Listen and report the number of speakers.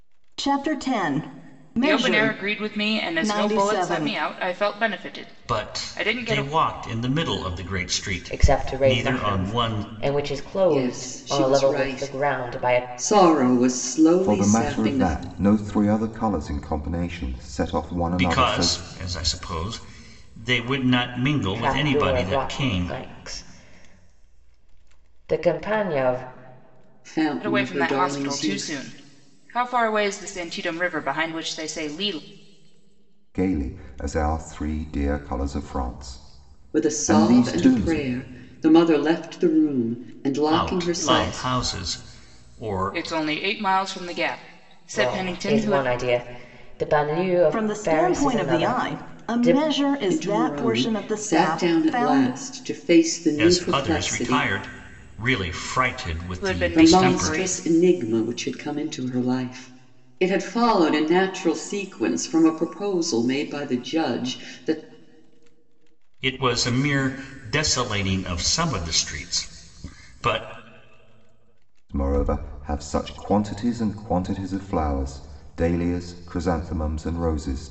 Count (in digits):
6